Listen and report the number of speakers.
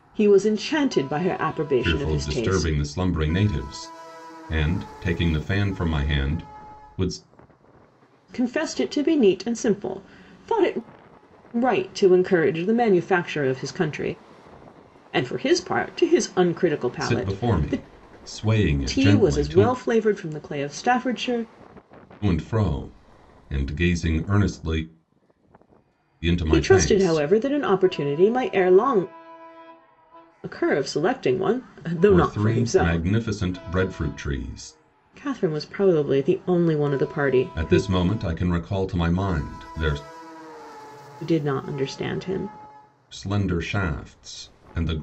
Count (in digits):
2